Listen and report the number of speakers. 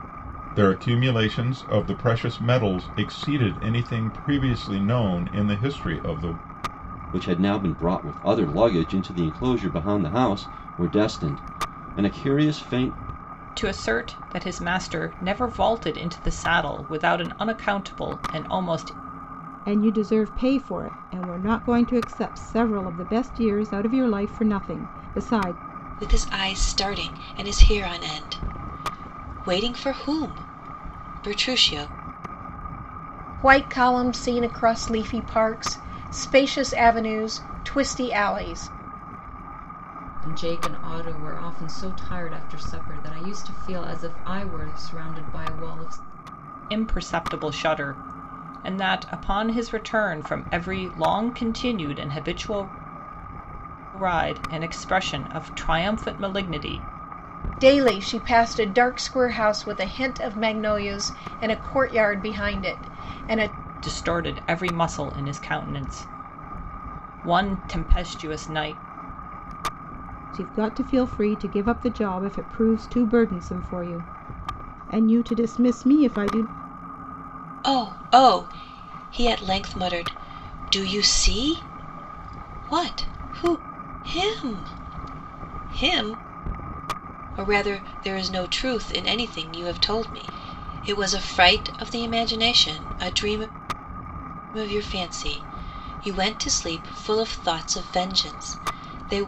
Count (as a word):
seven